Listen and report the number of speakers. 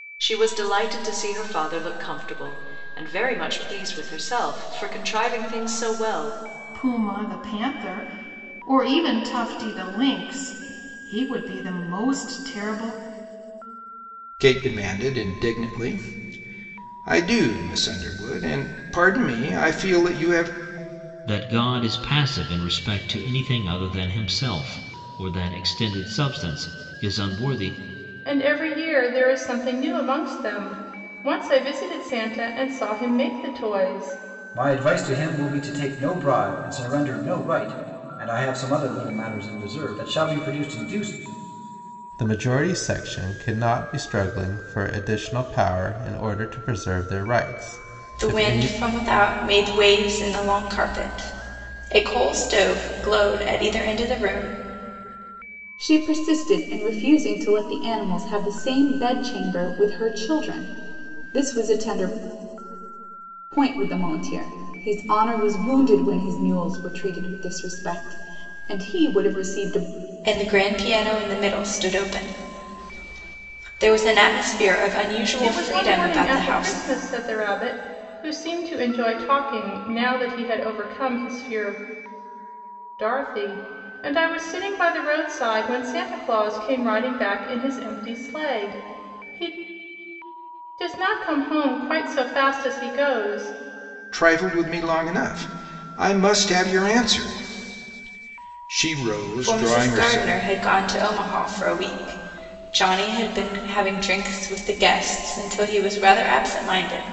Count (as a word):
nine